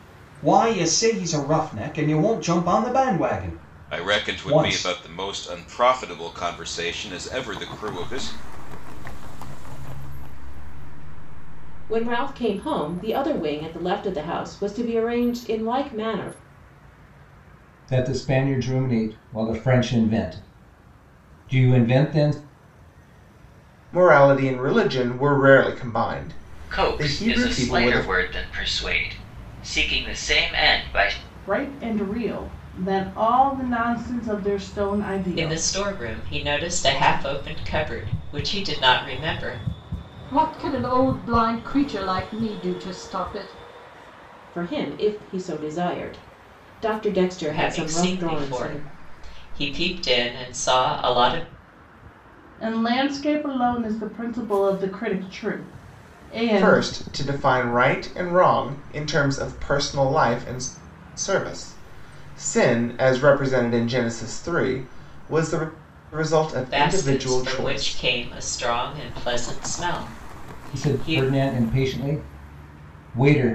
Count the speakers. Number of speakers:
10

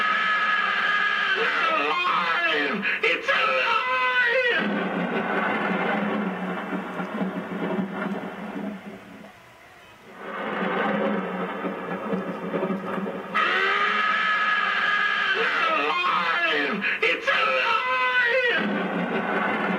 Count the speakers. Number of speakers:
0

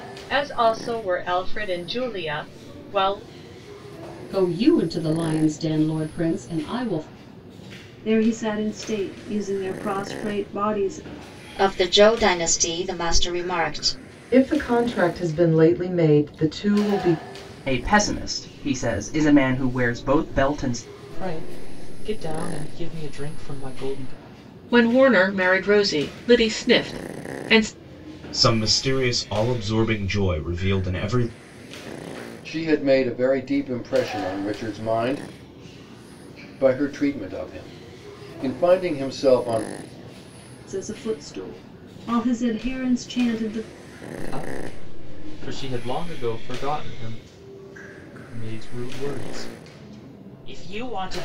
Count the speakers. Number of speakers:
10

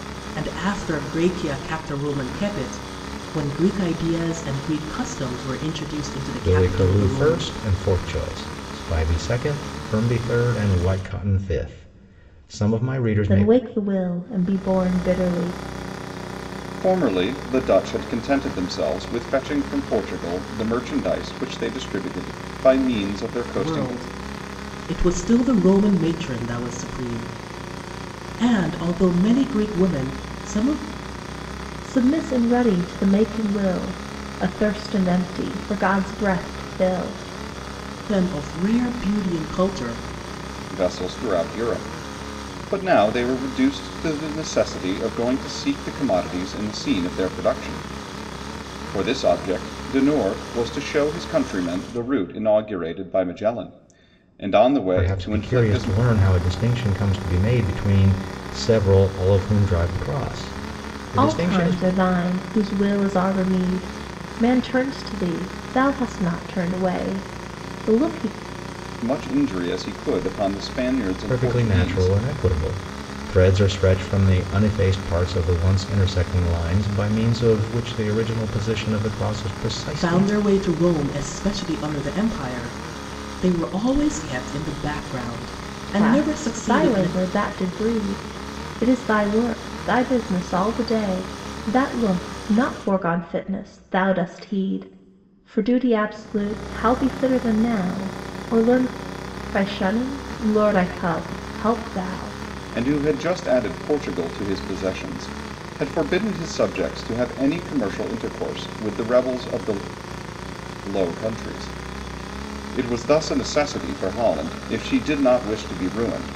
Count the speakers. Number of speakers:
4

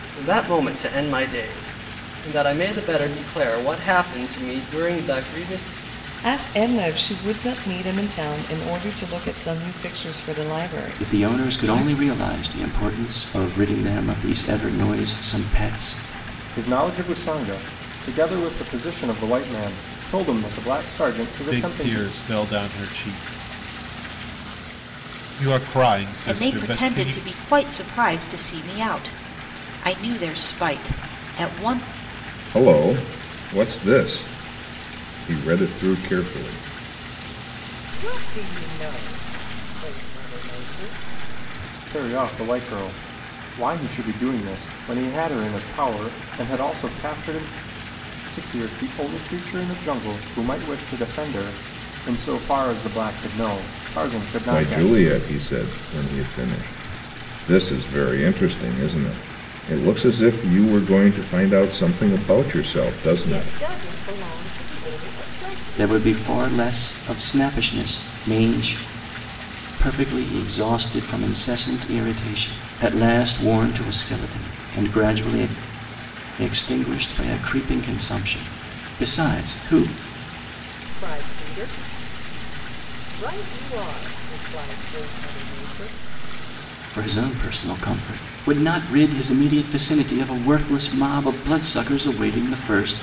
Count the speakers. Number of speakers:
8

